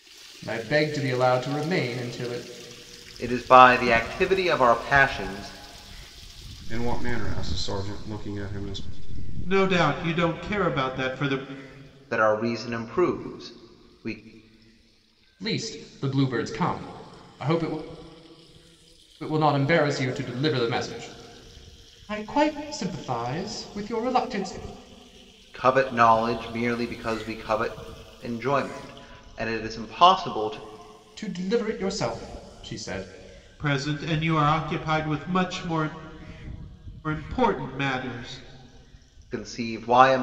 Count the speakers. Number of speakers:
4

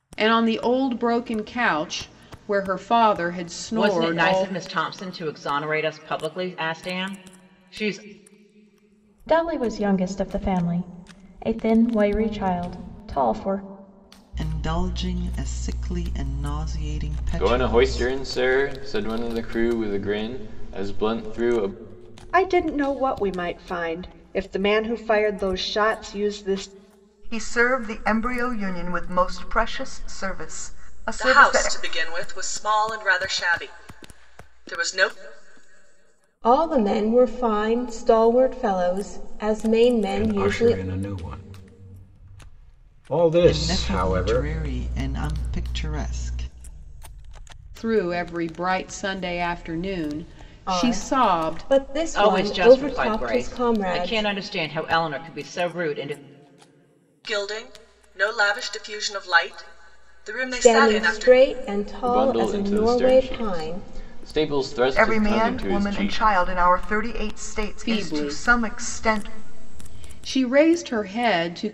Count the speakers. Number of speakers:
10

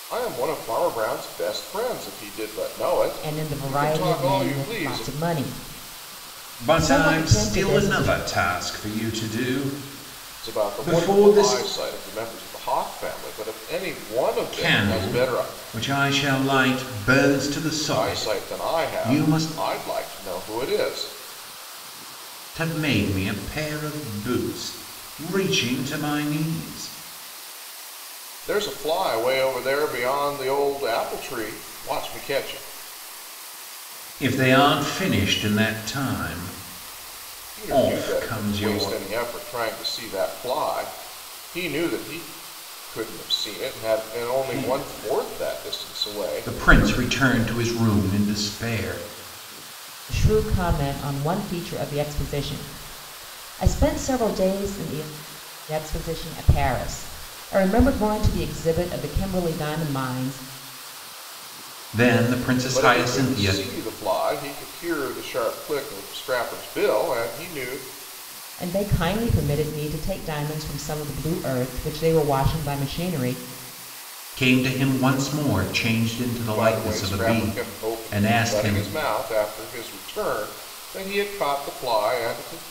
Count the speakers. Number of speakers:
3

